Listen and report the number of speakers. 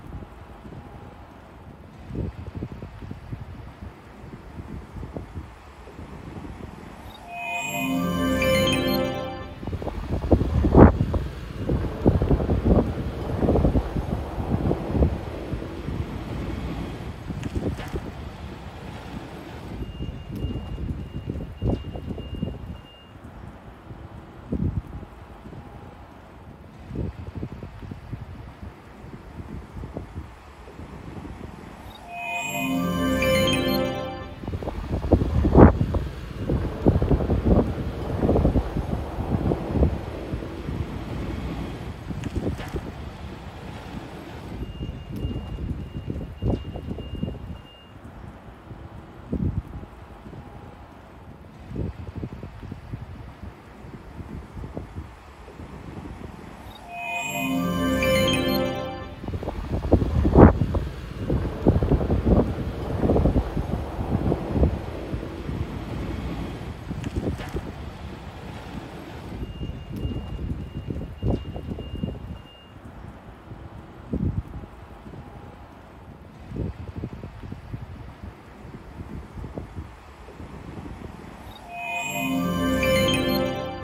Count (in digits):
0